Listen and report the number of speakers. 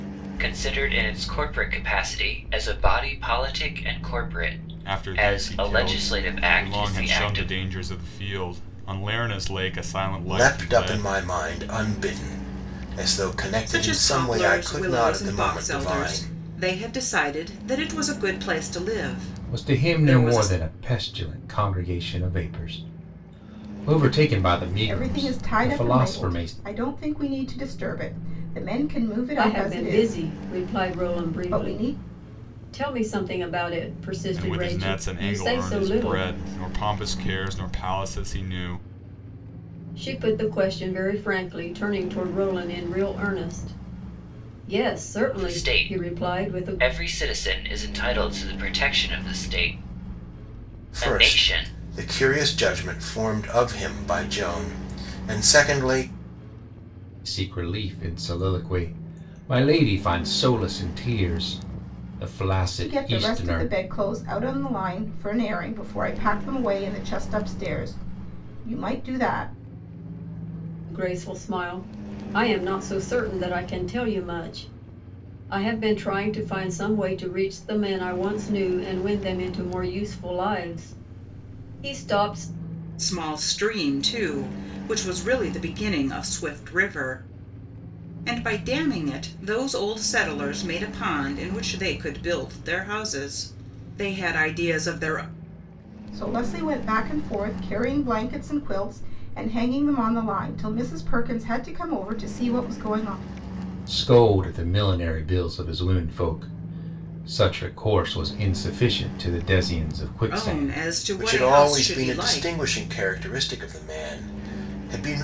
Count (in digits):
7